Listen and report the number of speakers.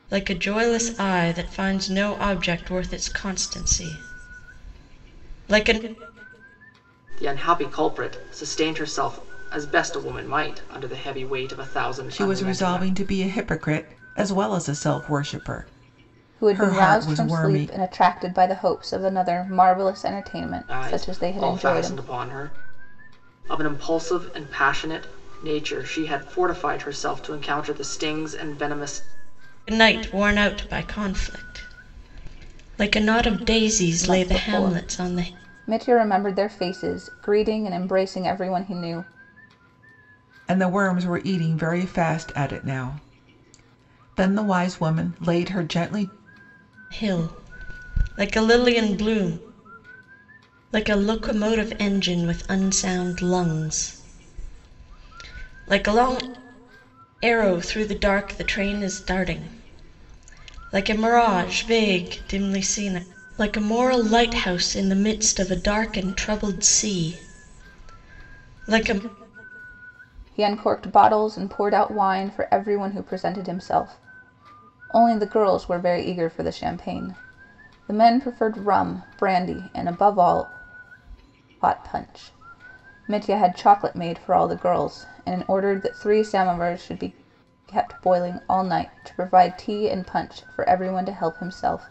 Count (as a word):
four